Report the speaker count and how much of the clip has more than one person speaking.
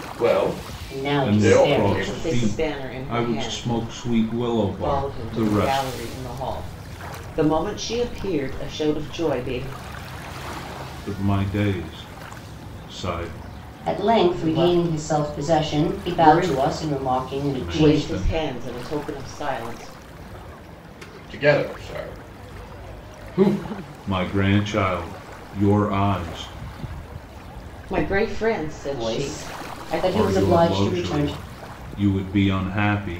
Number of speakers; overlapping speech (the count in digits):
4, about 29%